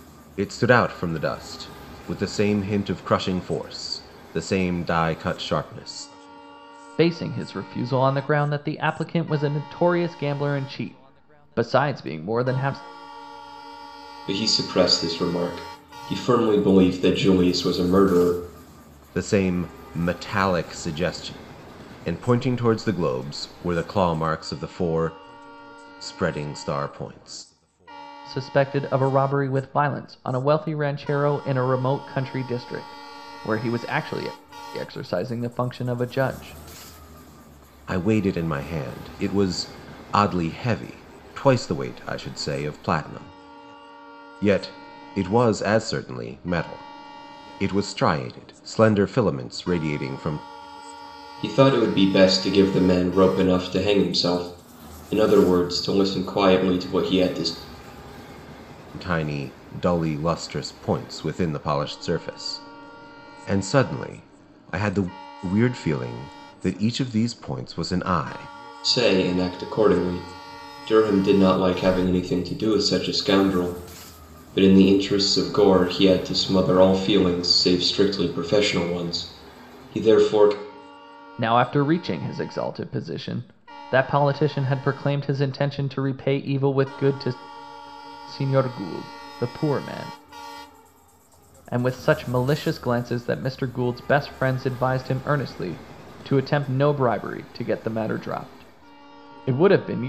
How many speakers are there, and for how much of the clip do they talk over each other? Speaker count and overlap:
3, no overlap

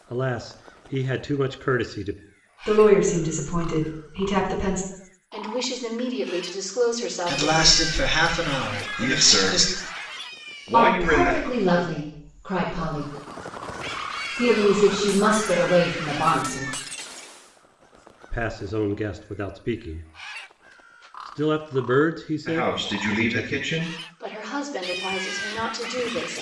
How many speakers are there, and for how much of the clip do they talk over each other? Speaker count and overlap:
6, about 12%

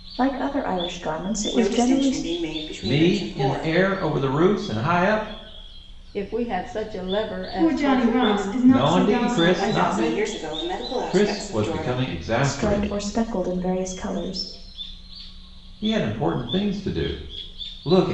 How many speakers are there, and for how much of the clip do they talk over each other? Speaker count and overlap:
5, about 31%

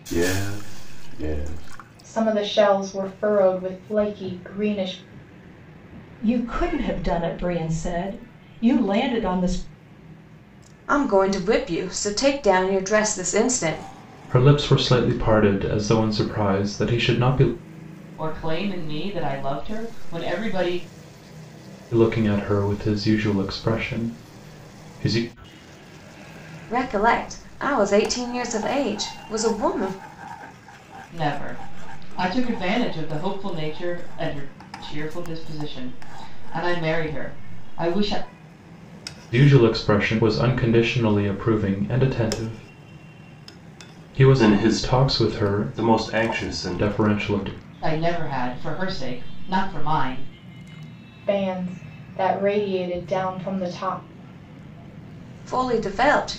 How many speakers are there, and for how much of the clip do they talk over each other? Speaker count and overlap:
6, no overlap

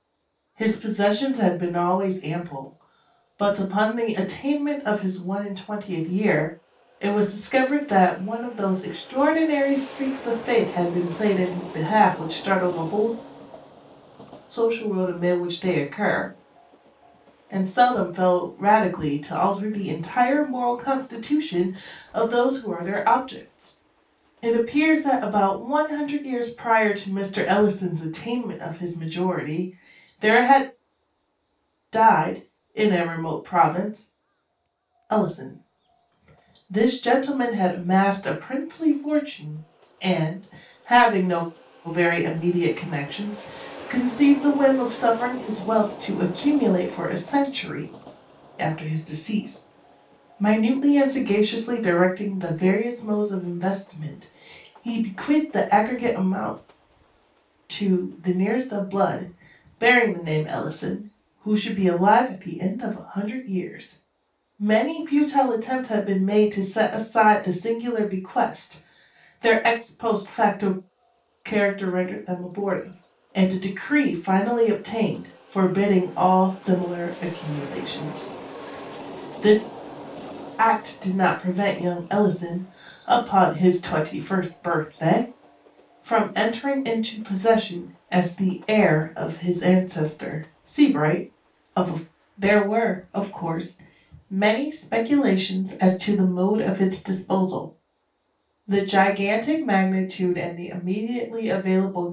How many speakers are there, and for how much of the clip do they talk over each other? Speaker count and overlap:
1, no overlap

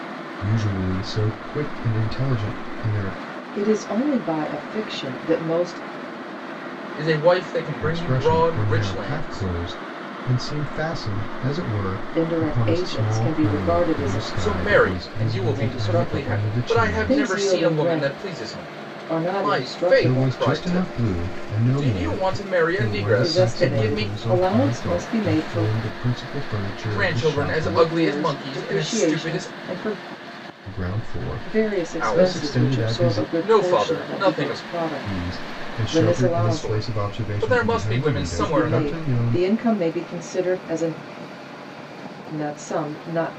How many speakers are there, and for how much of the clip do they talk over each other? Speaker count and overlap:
3, about 55%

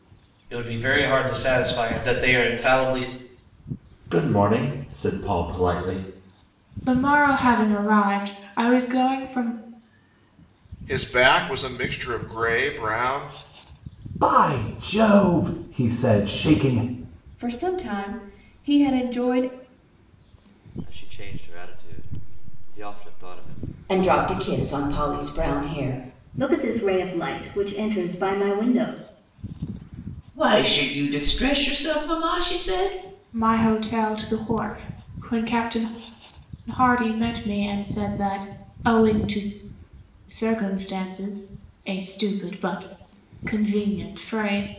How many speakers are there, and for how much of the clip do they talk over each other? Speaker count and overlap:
10, no overlap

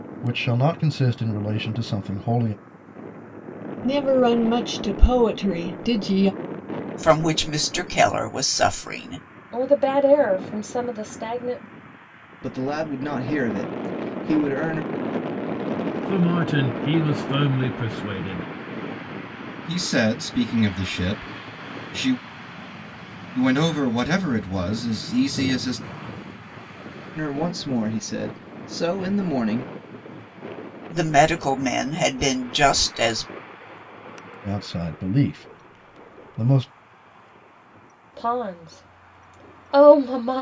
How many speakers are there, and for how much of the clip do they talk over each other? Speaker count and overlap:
7, no overlap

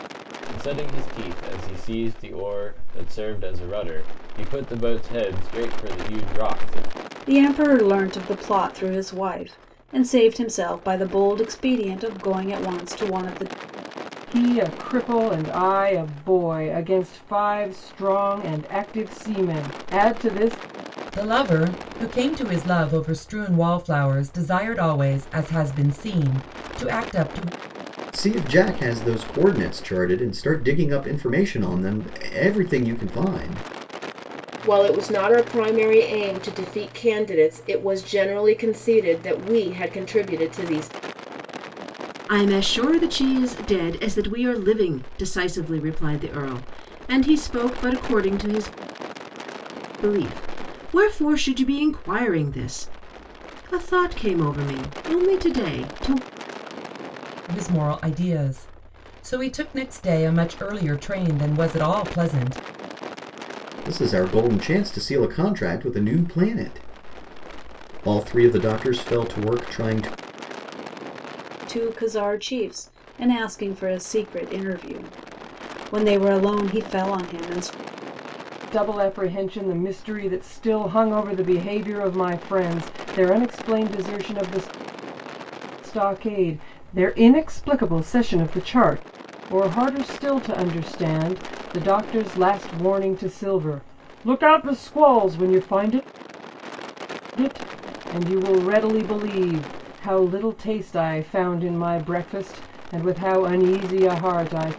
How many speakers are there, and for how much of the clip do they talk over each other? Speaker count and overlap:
7, no overlap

